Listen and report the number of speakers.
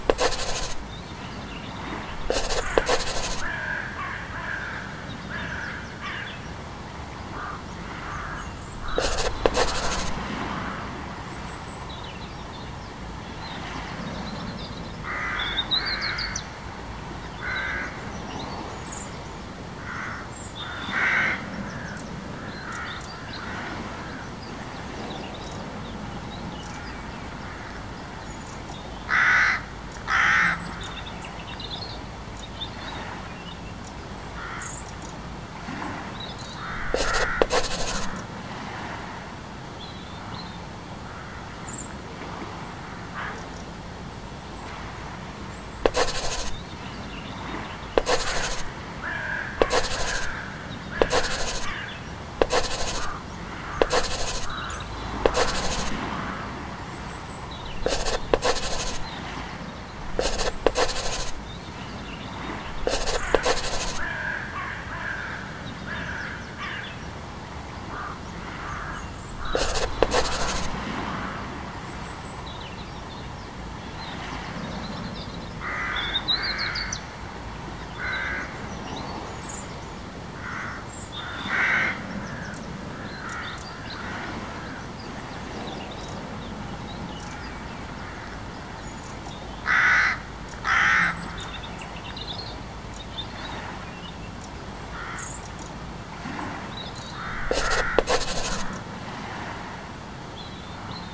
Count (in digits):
0